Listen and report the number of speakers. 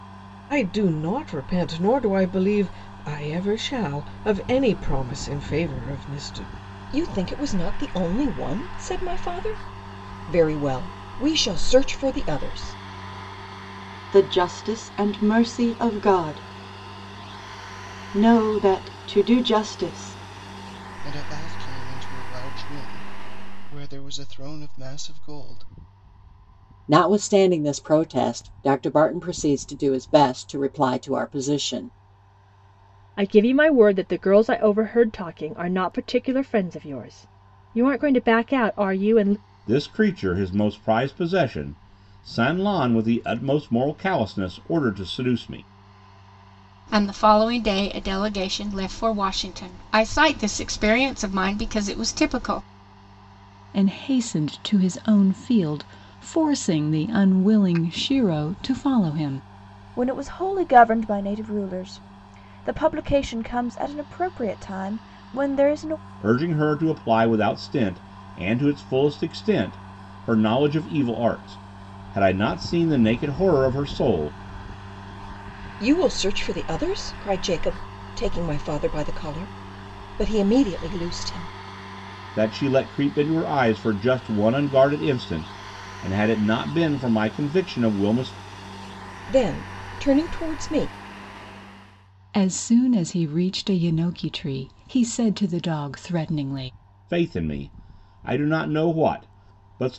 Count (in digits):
10